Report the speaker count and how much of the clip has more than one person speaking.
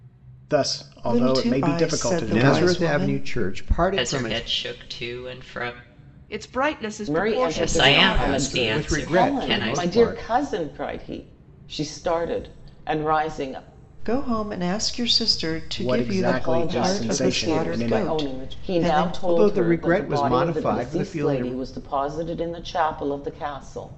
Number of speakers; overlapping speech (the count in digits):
6, about 49%